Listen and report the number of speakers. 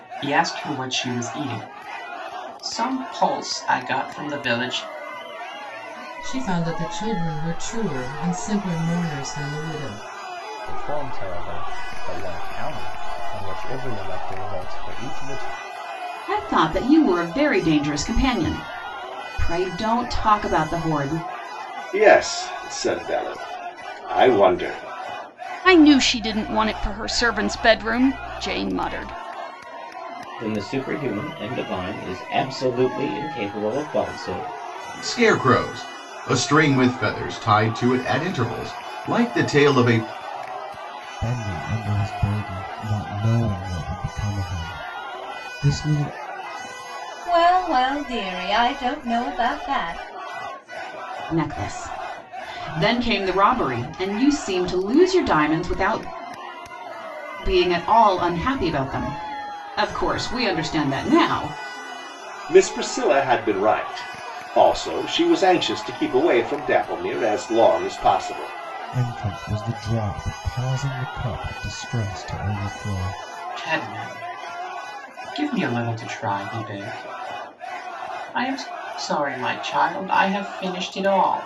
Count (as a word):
ten